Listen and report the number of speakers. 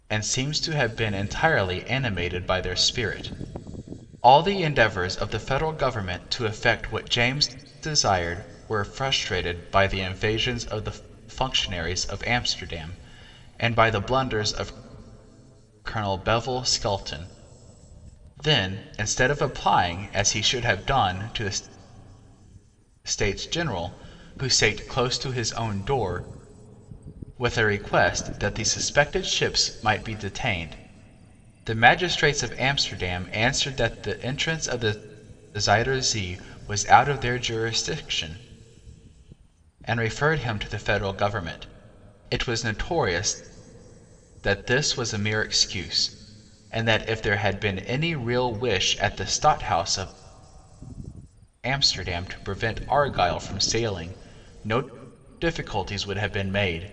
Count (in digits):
1